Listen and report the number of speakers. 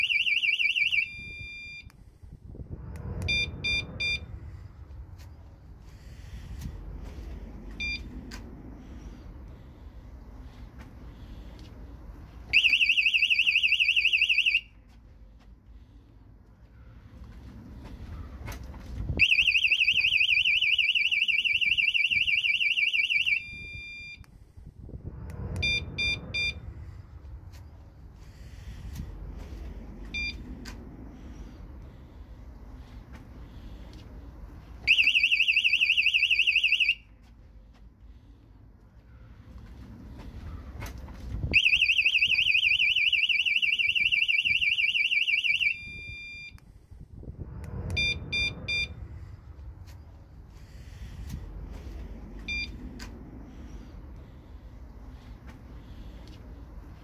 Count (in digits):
0